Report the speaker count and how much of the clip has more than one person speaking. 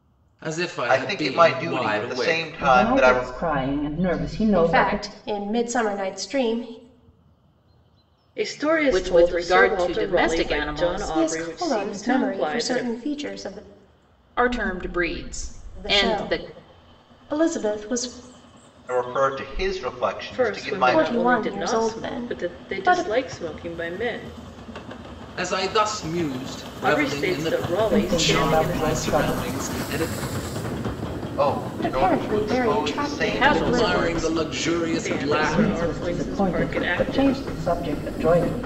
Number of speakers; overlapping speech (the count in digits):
6, about 47%